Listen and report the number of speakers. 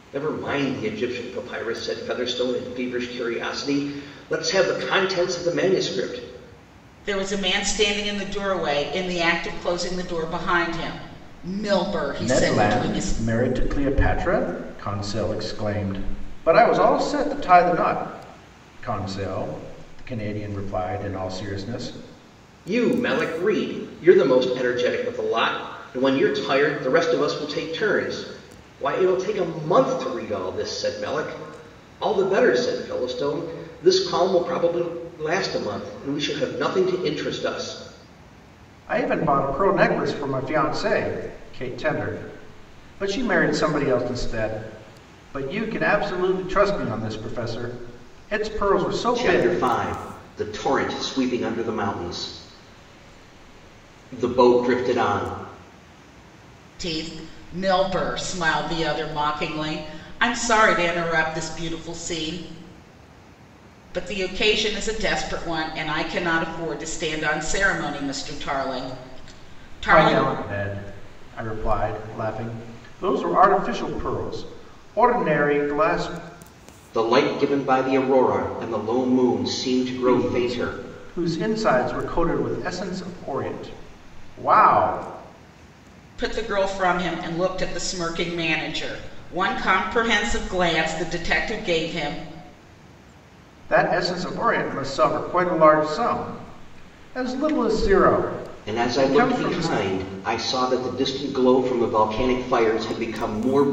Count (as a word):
three